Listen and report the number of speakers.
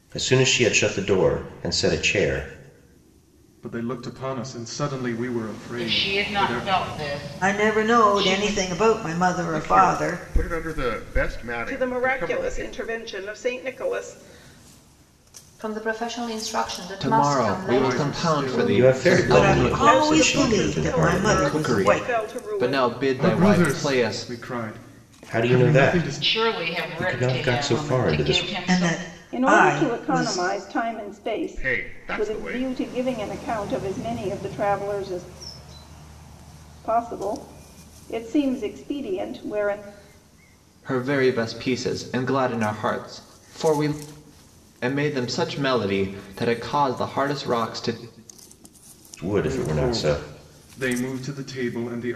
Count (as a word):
eight